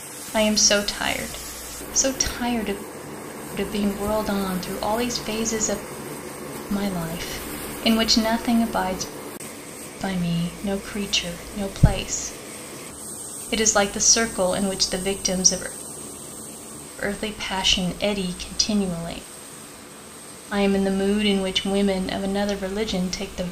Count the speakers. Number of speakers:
one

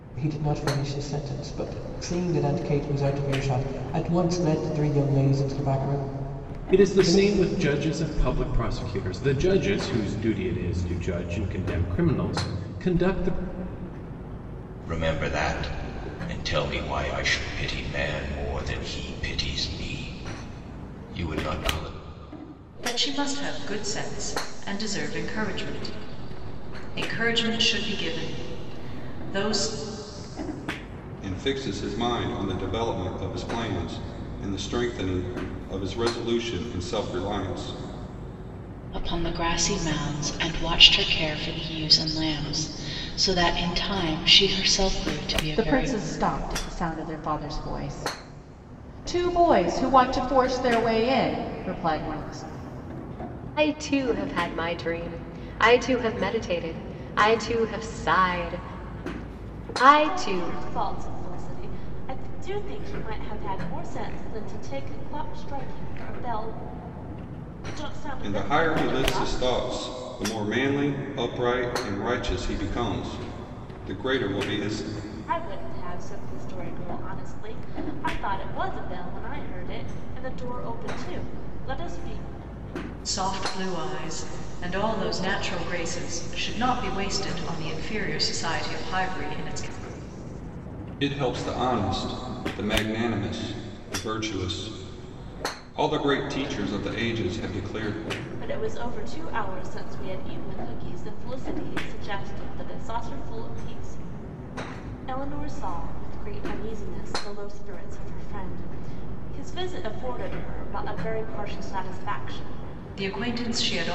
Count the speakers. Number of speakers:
nine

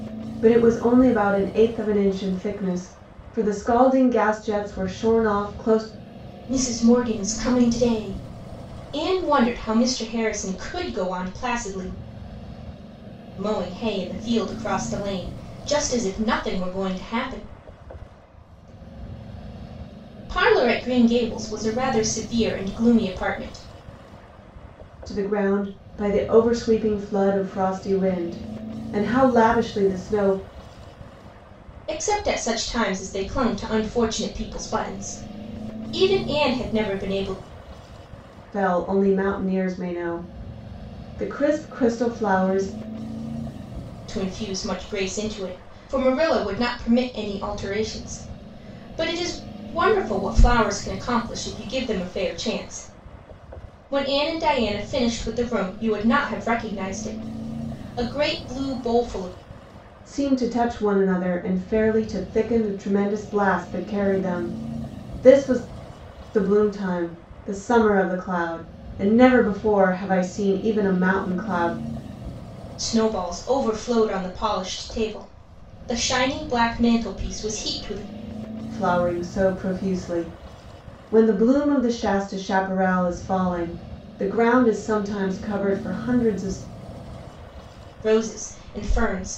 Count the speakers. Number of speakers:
two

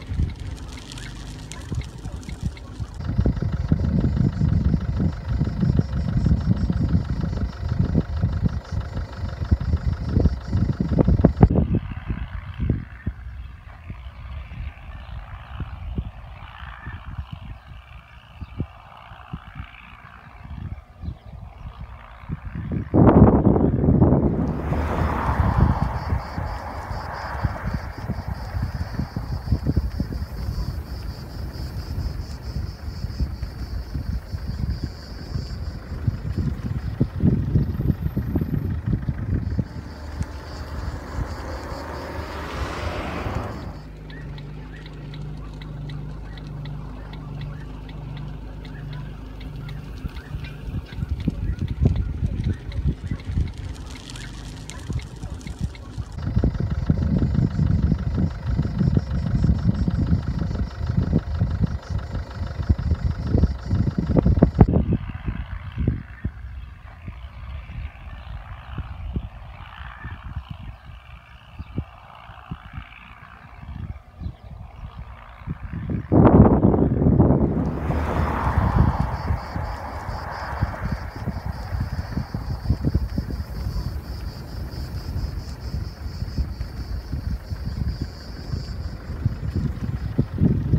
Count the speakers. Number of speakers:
zero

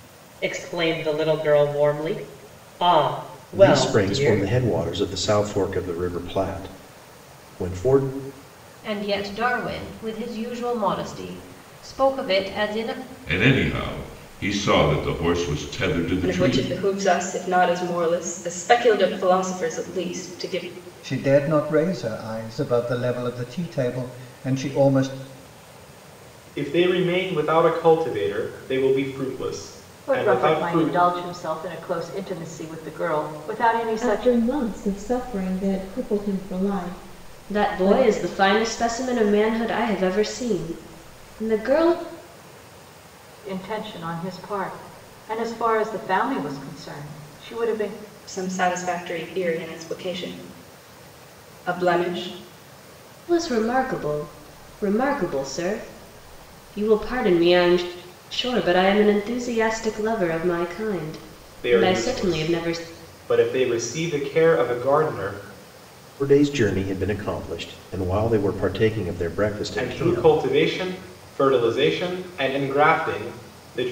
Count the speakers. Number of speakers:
ten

